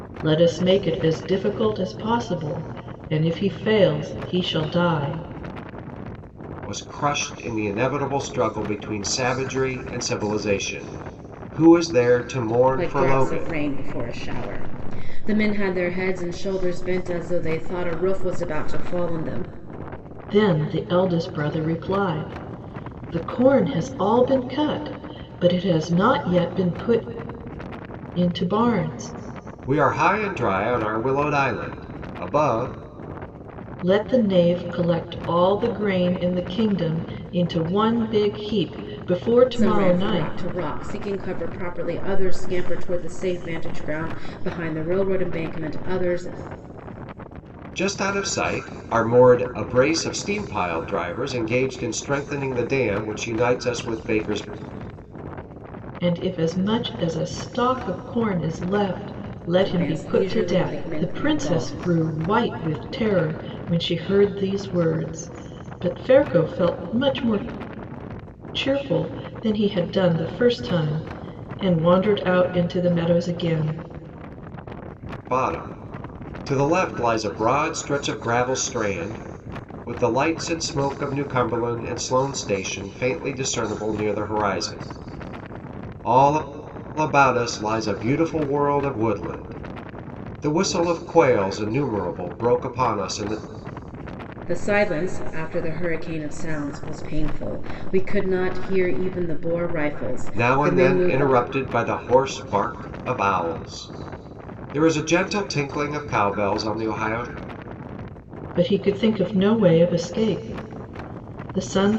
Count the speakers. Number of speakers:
three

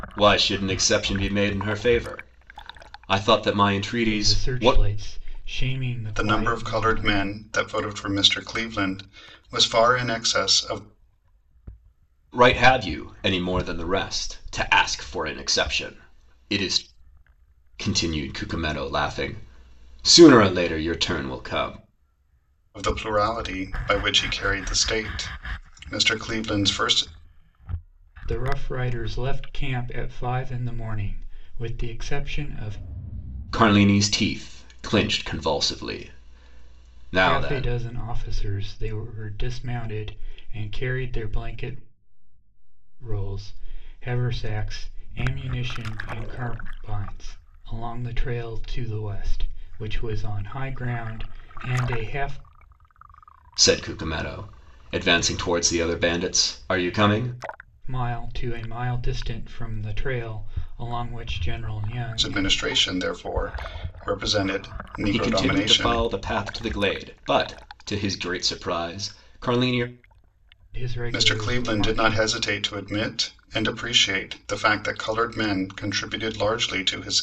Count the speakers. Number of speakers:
three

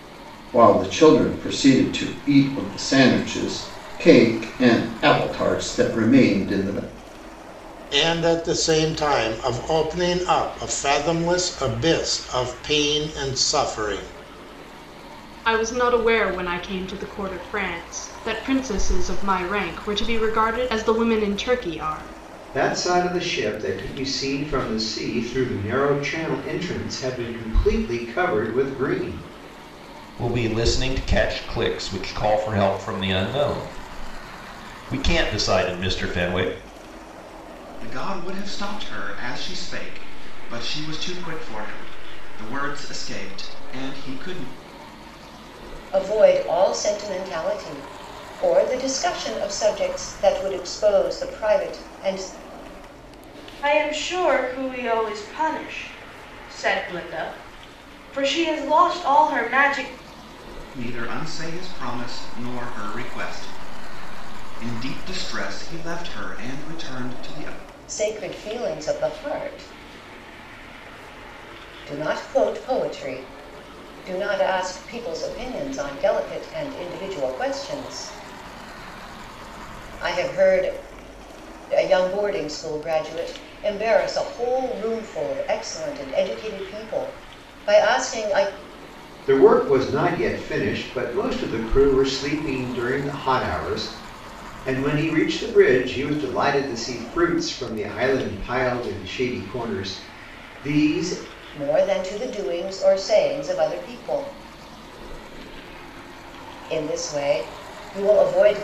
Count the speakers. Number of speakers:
eight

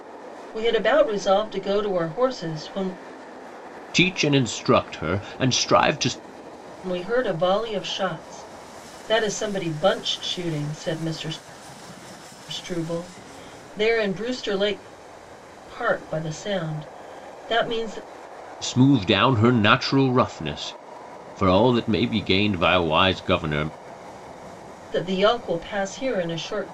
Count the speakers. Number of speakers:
two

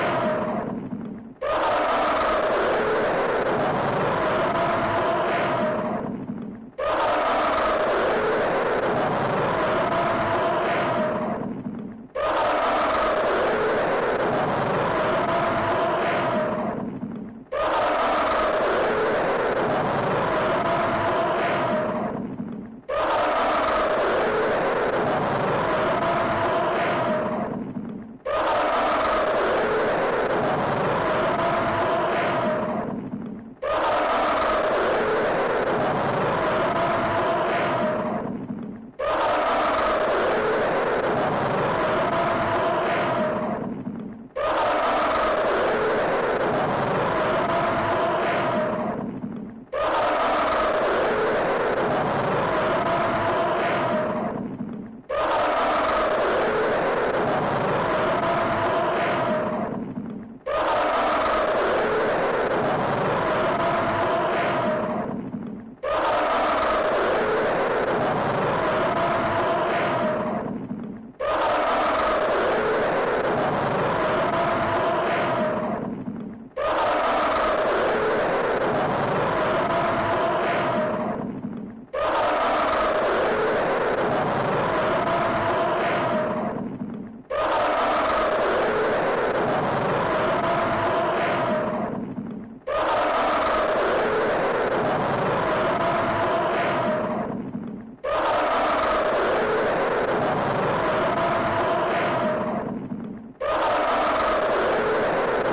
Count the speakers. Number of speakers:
zero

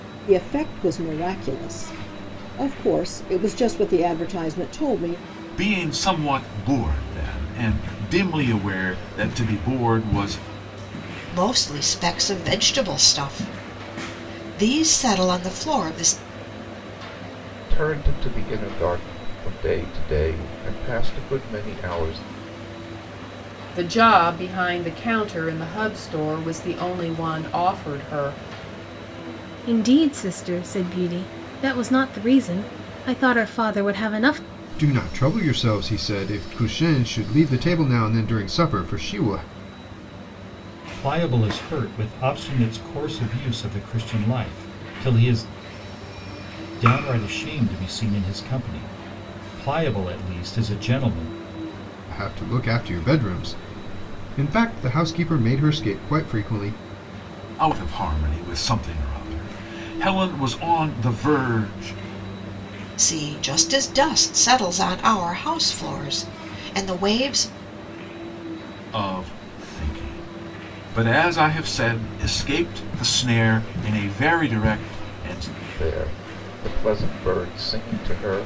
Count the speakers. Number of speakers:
eight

